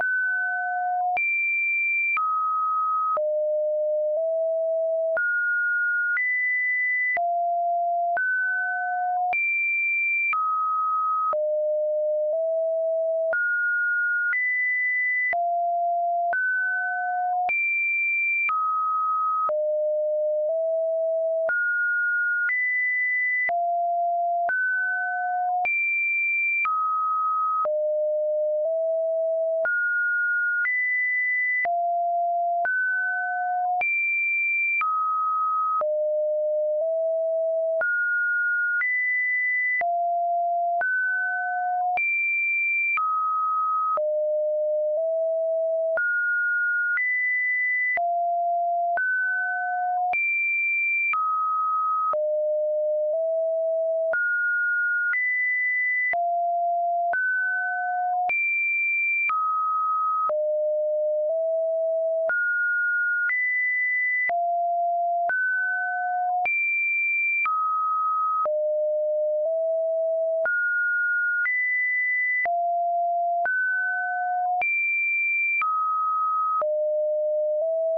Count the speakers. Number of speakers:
zero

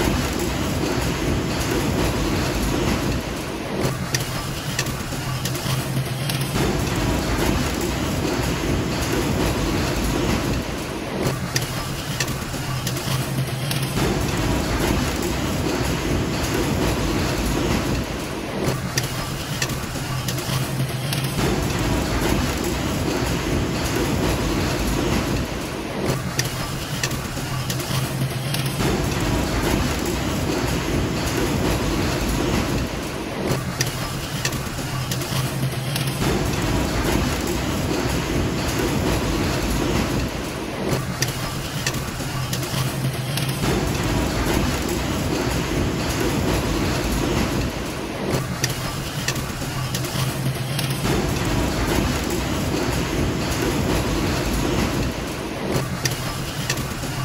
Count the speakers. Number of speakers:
zero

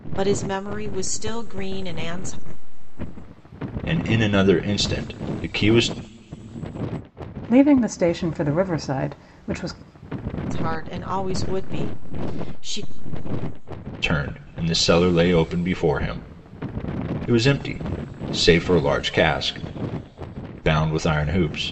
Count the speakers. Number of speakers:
three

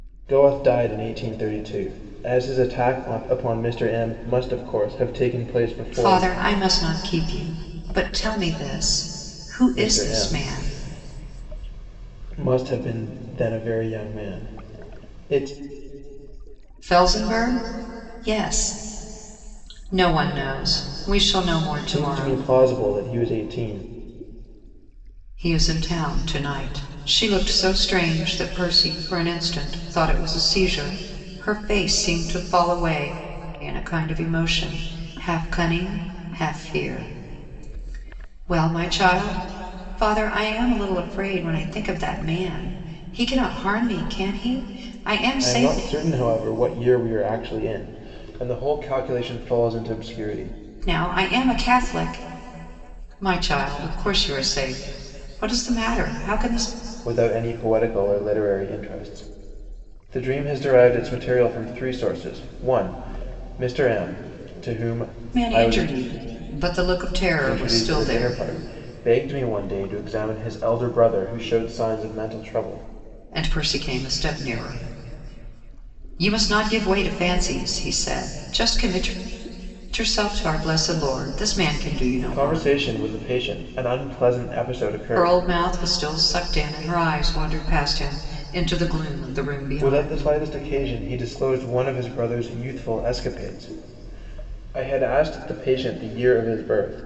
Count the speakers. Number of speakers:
two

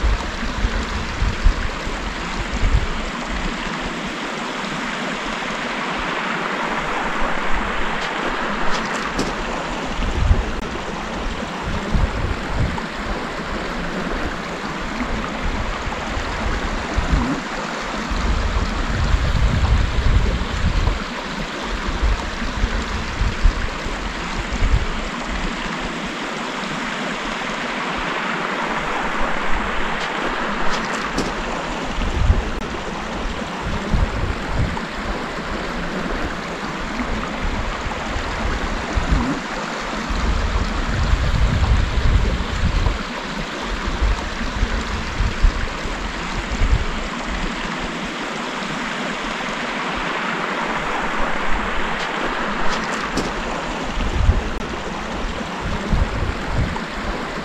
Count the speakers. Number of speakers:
zero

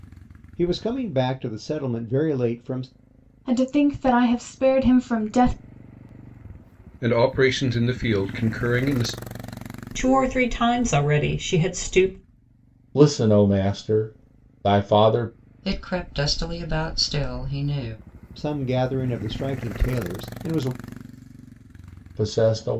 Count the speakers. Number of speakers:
six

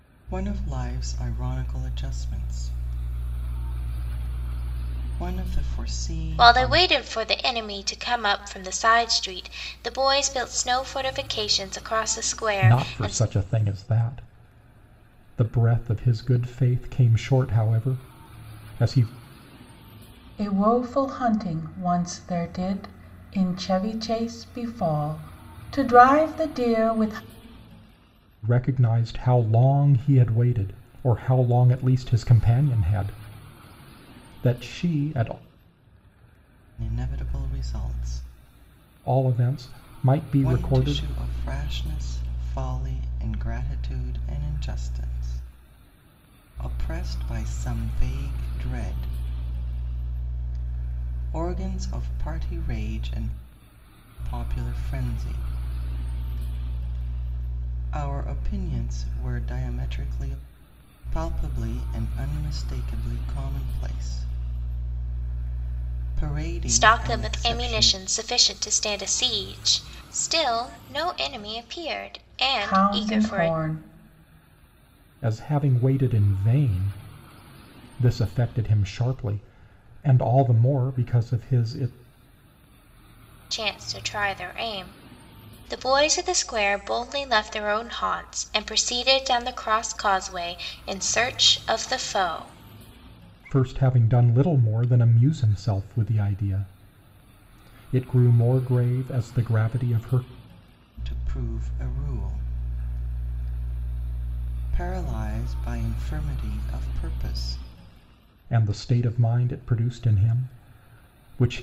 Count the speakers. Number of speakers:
four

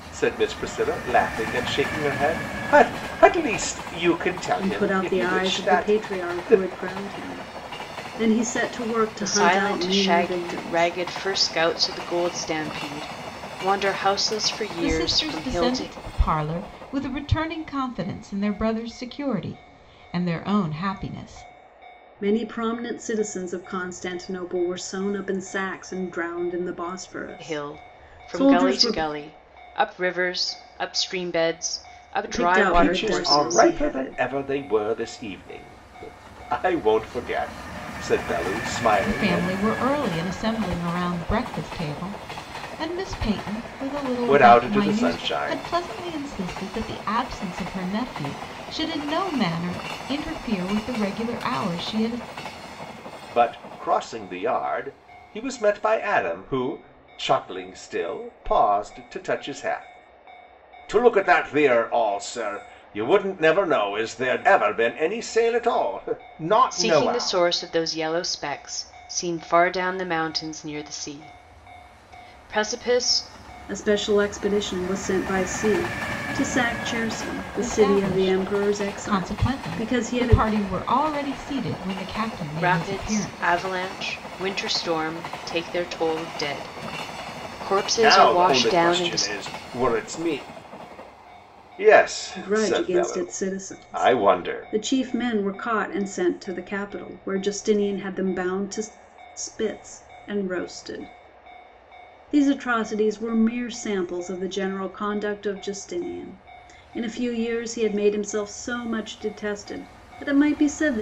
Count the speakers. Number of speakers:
four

